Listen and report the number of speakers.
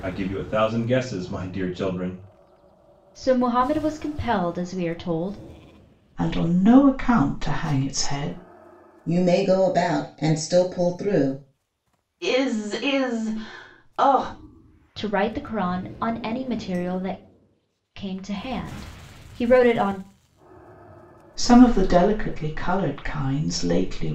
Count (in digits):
5